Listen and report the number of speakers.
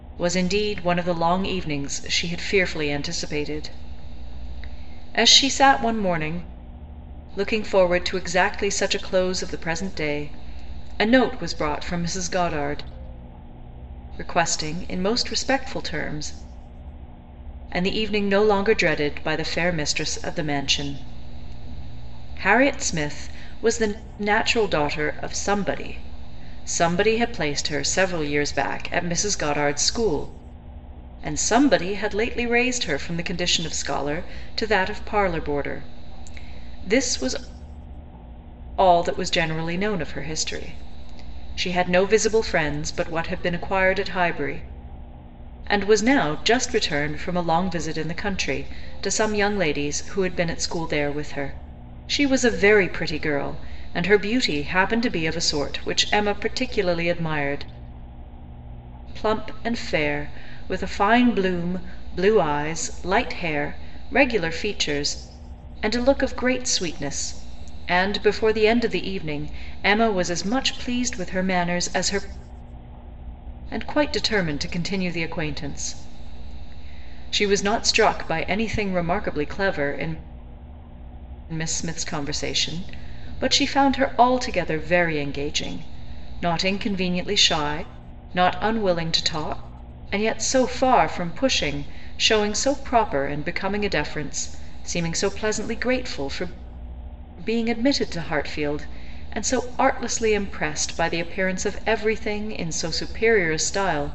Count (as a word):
one